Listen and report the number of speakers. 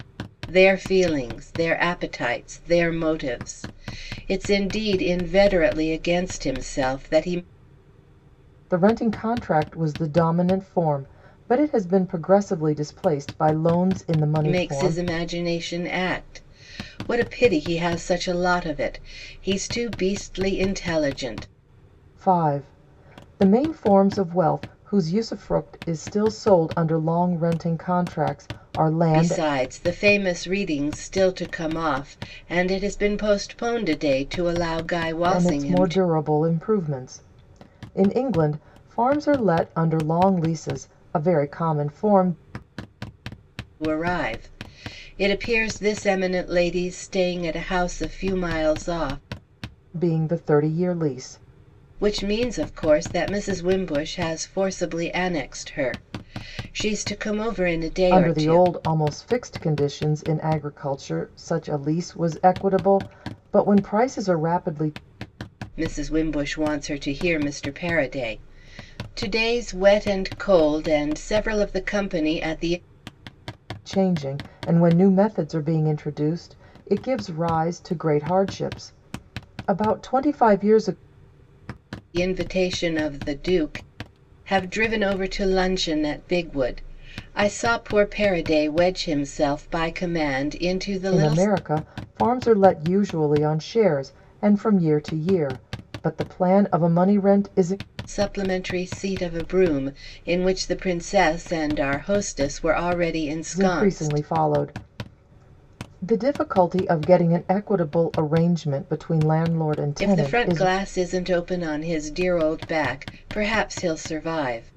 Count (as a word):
two